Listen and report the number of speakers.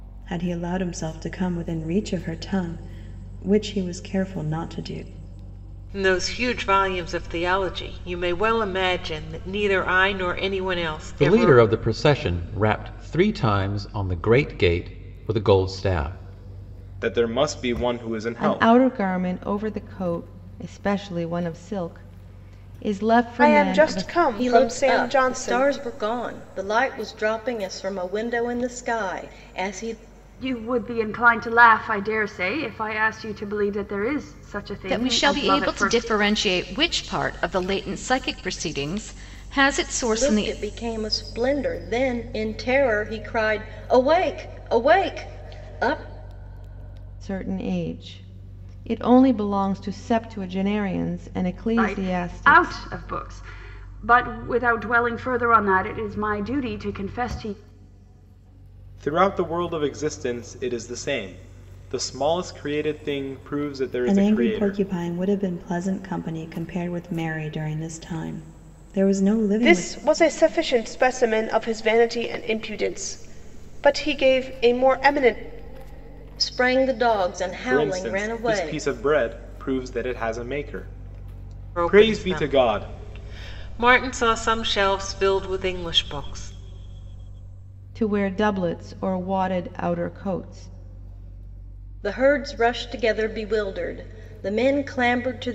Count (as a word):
nine